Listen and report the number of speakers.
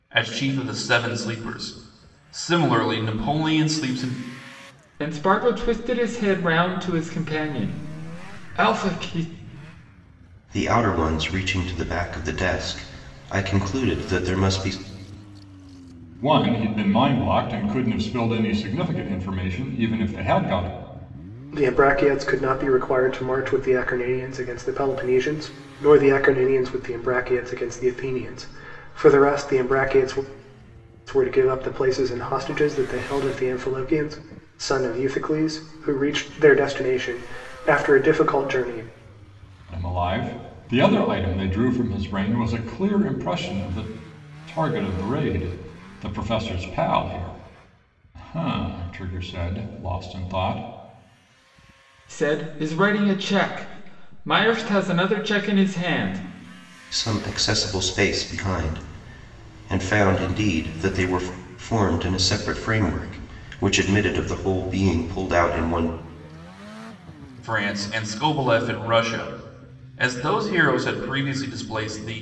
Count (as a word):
five